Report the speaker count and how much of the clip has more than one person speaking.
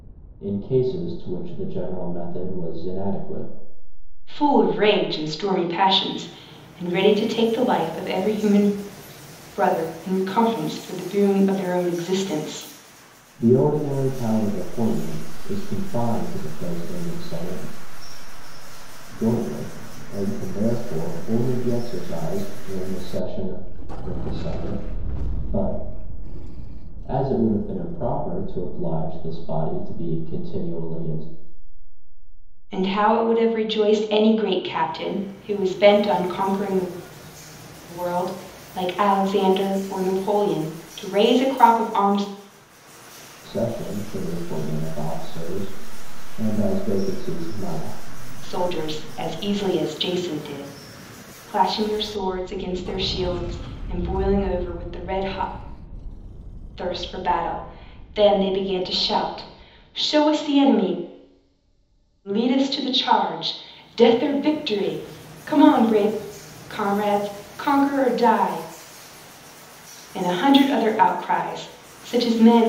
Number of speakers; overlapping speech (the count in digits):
2, no overlap